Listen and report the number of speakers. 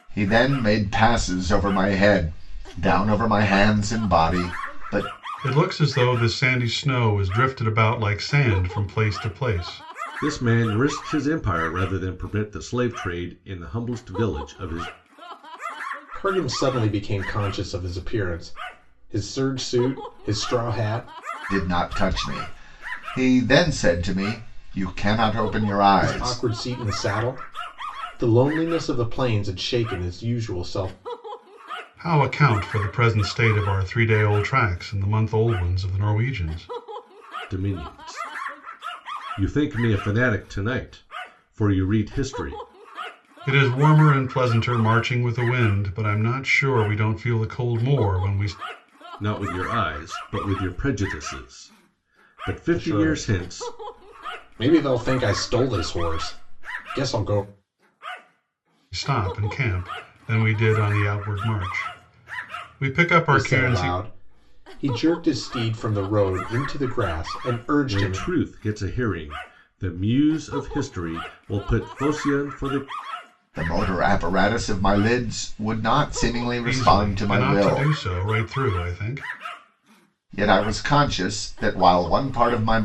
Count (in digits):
4